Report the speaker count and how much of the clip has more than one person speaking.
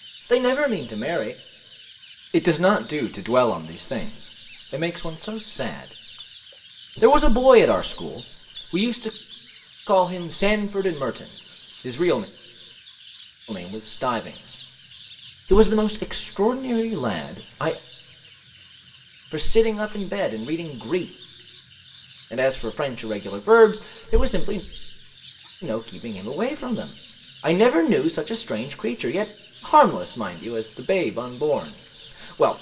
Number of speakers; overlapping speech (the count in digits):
1, no overlap